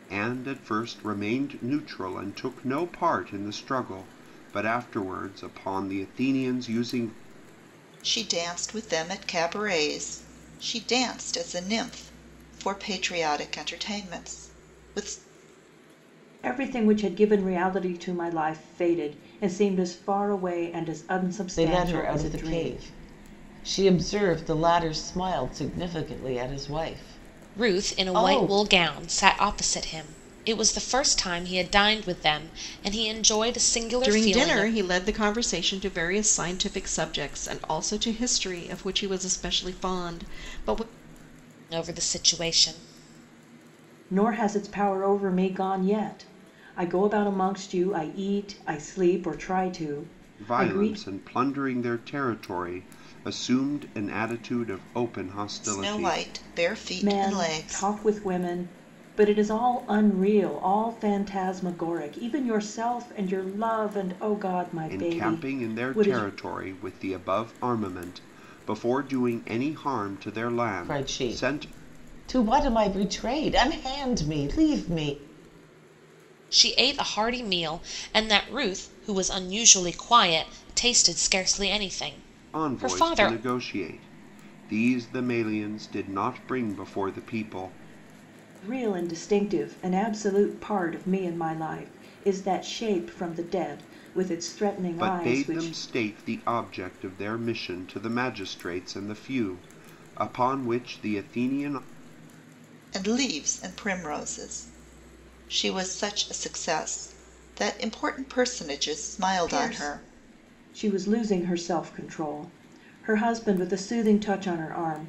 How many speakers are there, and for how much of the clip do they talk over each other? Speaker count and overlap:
6, about 8%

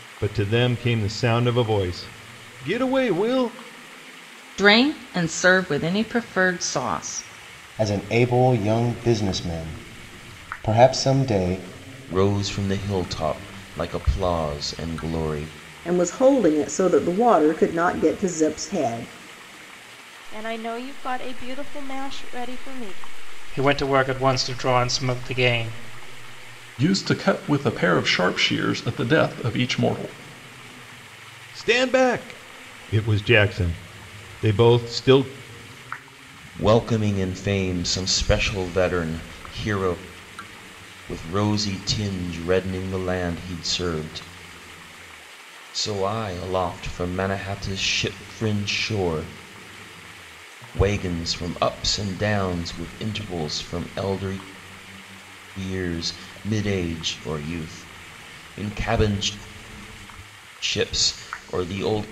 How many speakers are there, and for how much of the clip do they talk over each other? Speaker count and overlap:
8, no overlap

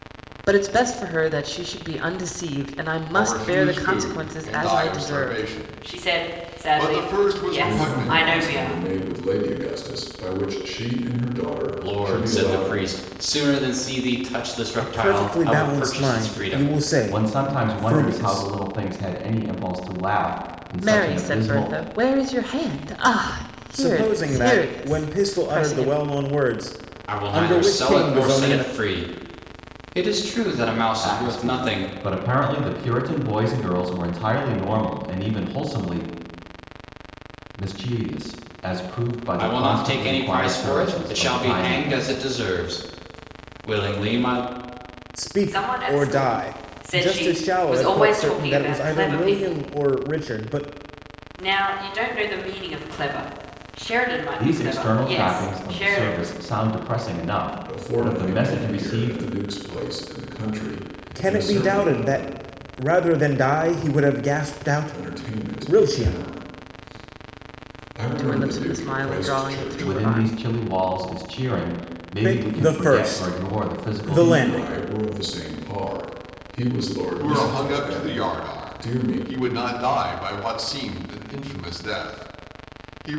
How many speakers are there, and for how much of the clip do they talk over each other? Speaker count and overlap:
7, about 43%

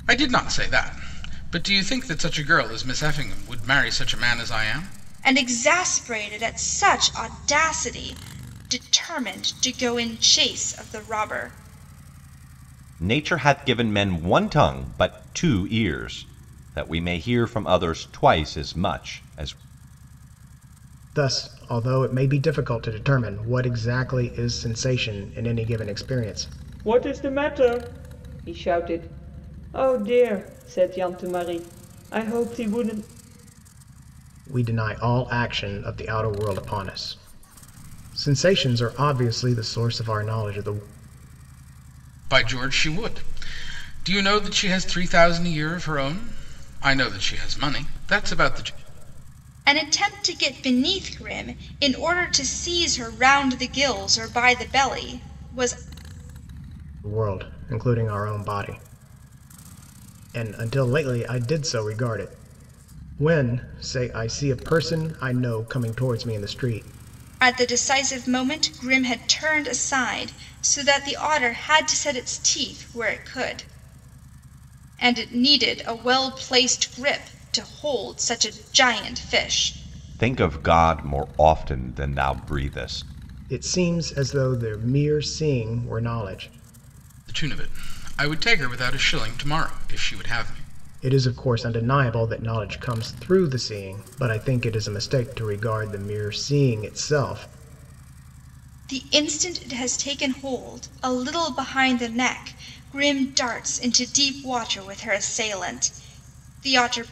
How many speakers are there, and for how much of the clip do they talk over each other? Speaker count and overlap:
5, no overlap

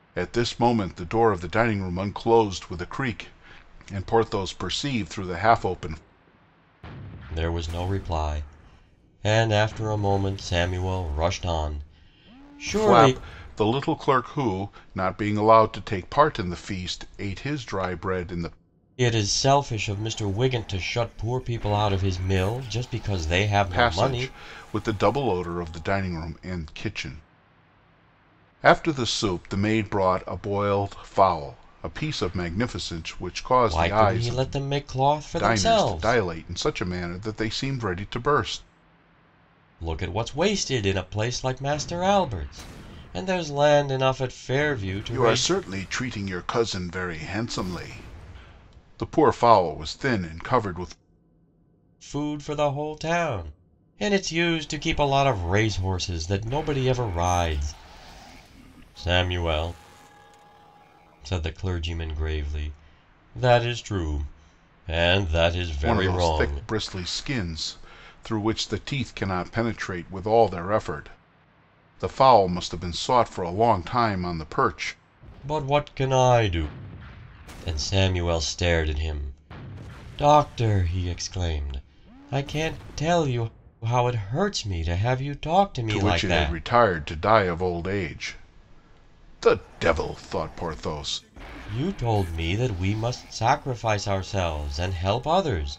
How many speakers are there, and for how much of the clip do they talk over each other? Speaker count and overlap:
2, about 5%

